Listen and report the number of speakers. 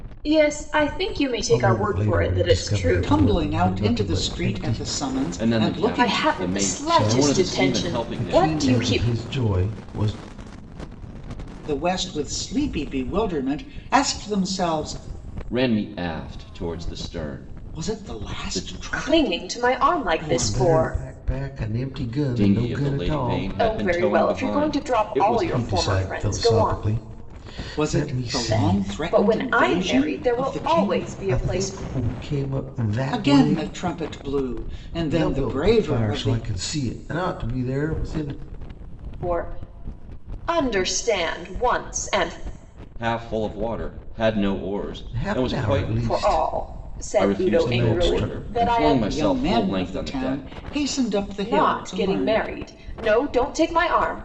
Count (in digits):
4